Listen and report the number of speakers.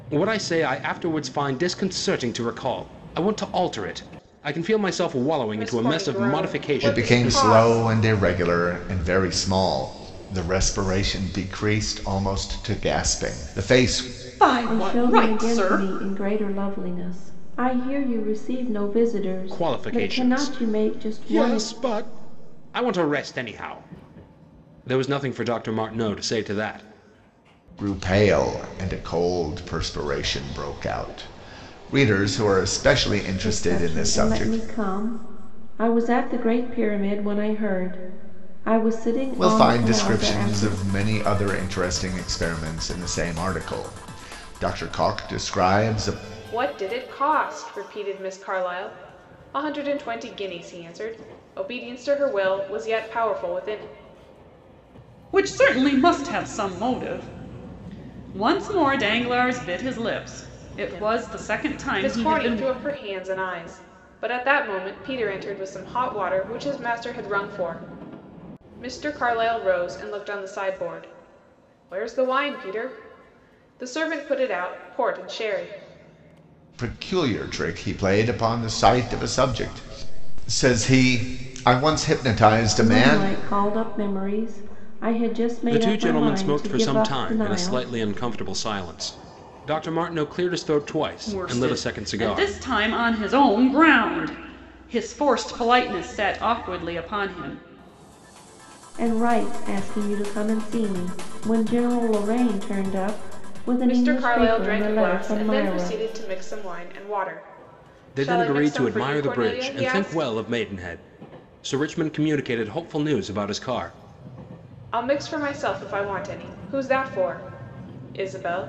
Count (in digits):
5